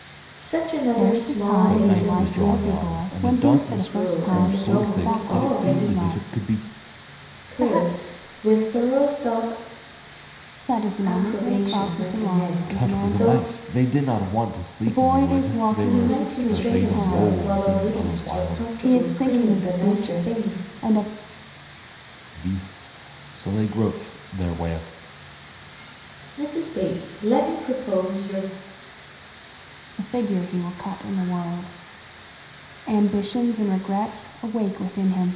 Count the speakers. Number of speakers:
3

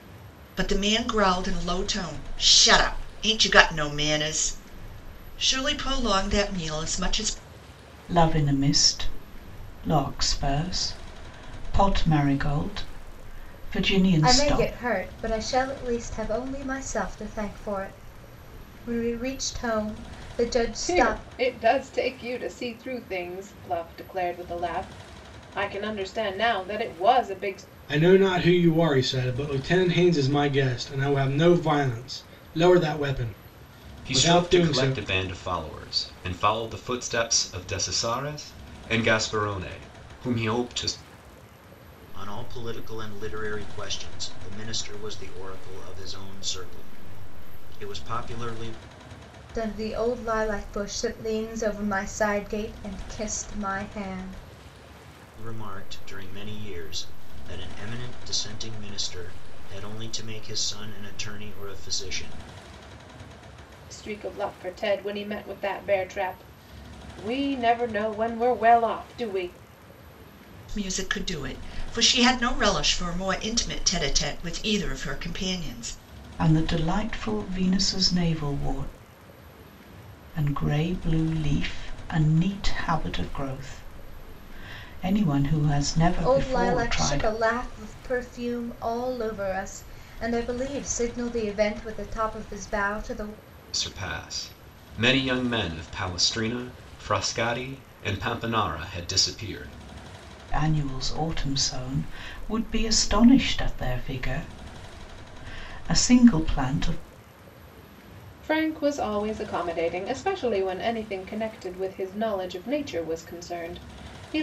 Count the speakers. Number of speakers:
7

